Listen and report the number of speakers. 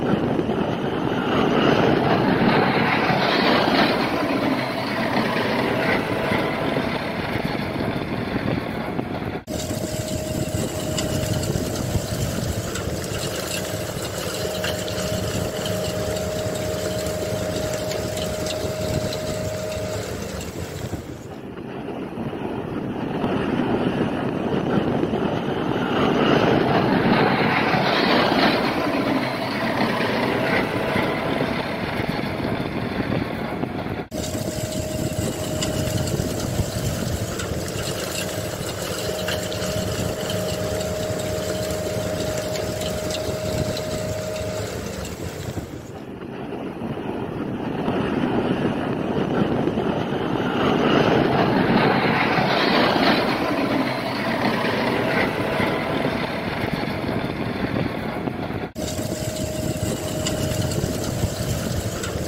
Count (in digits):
0